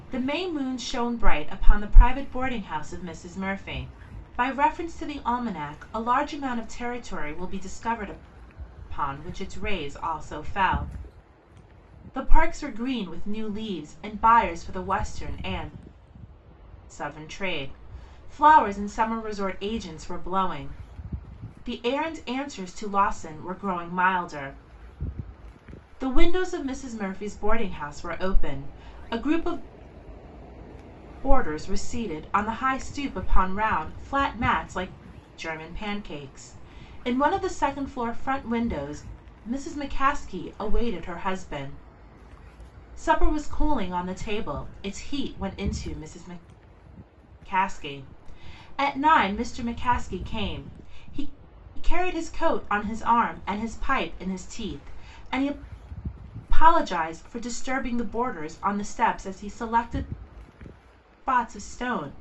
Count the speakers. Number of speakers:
1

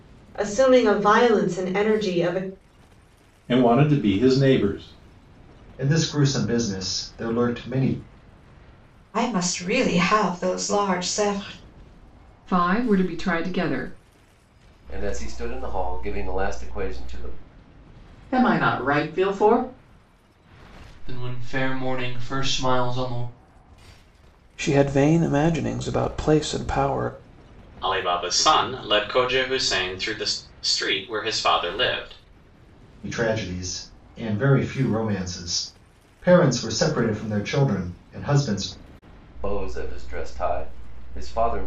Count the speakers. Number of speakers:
10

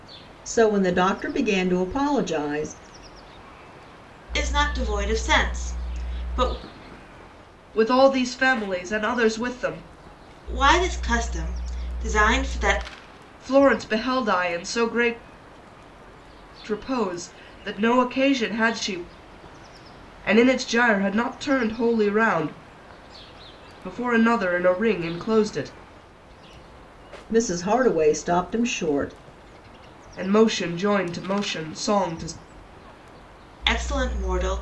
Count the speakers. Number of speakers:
3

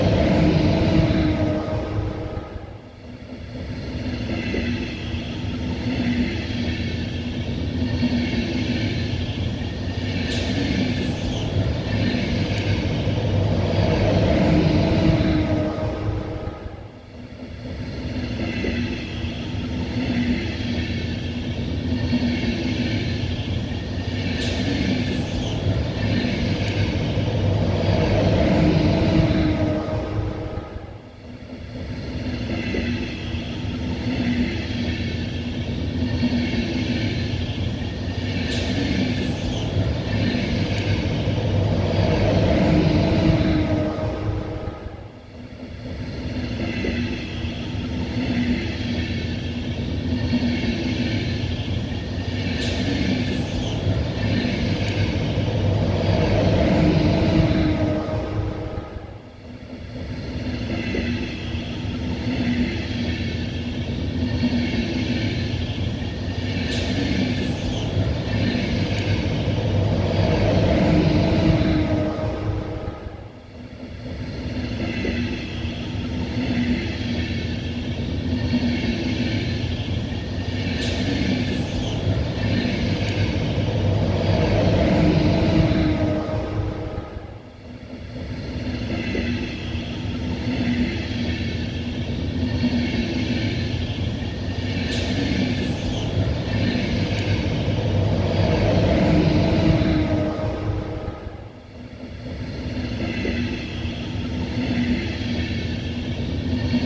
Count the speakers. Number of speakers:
0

